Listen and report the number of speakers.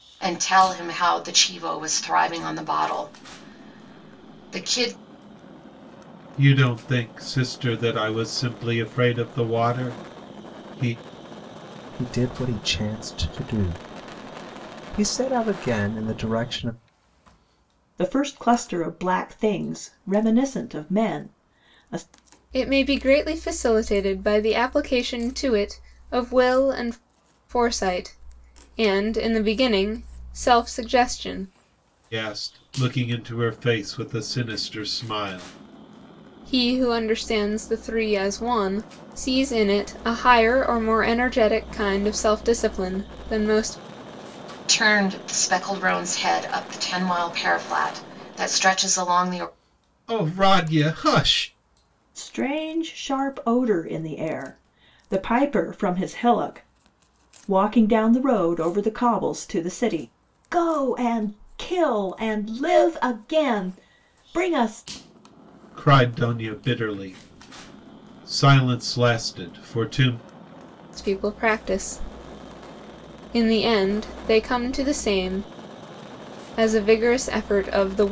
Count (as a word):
five